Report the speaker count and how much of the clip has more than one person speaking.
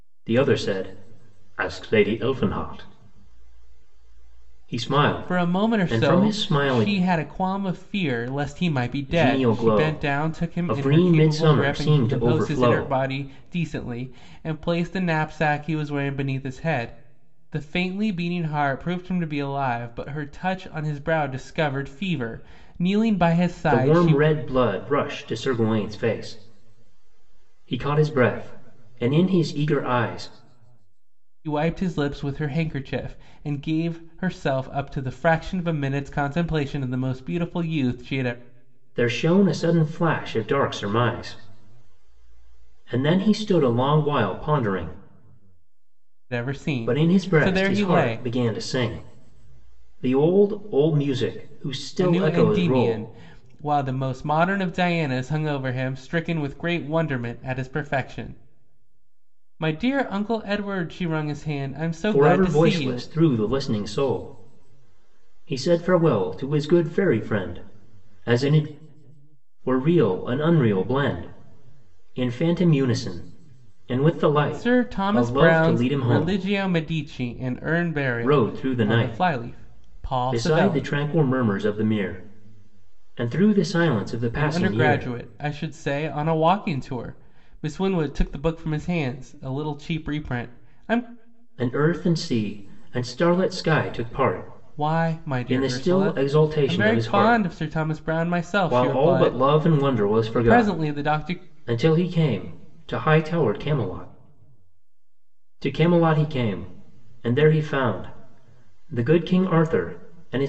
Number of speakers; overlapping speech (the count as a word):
two, about 19%